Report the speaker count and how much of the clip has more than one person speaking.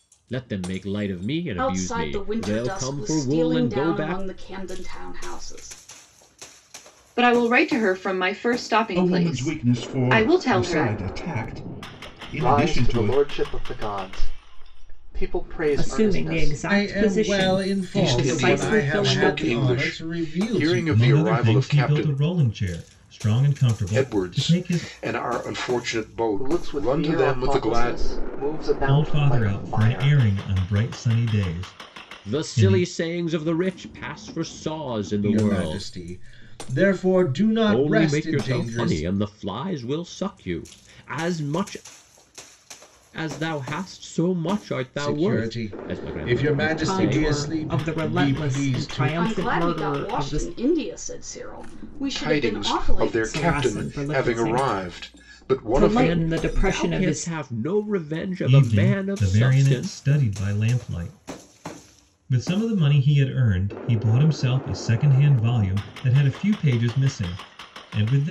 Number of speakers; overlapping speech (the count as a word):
nine, about 45%